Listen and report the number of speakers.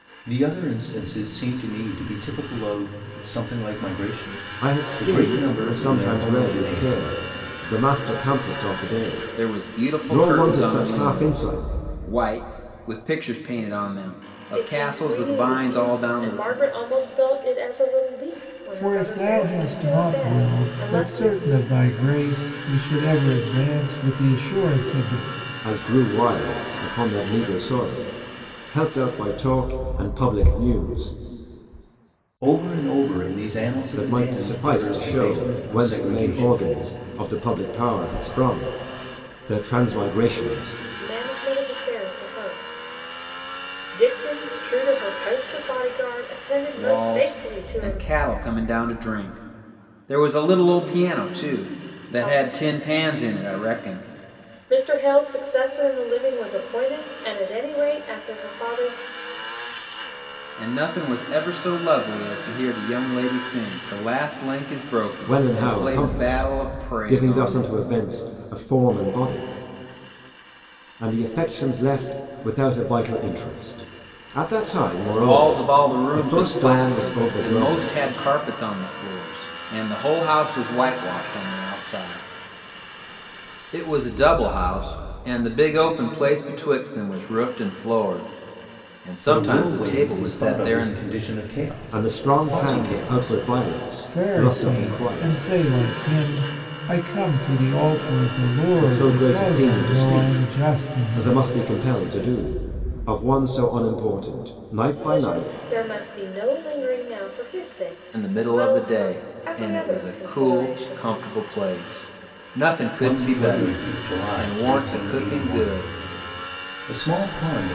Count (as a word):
five